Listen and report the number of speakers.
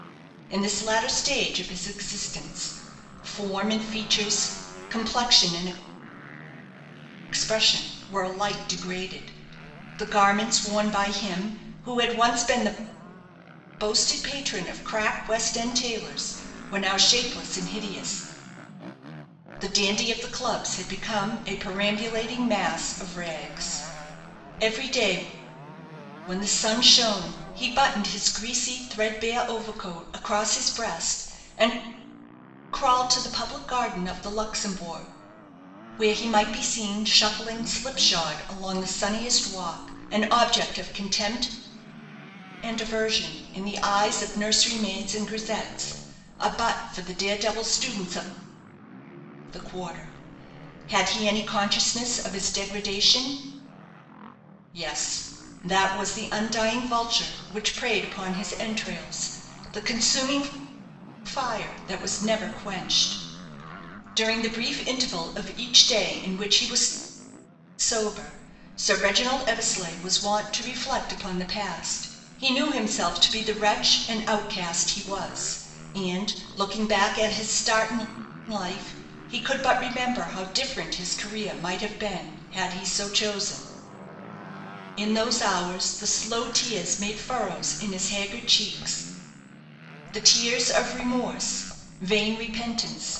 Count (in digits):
1